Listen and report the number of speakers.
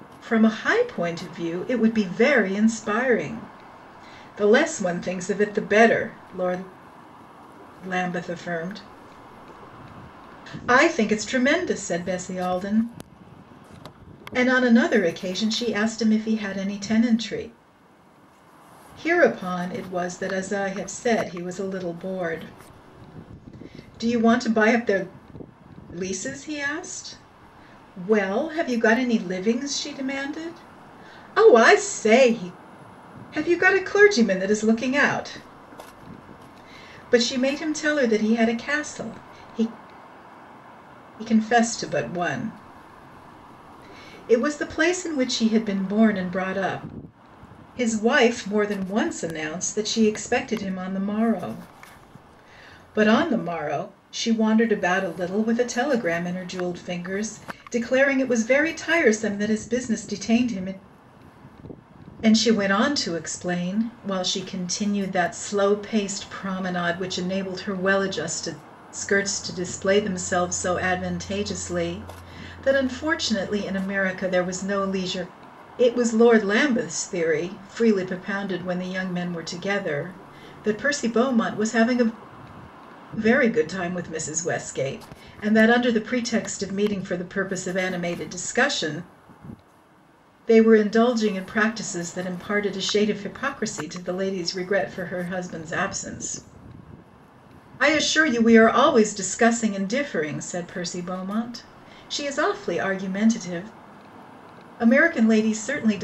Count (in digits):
1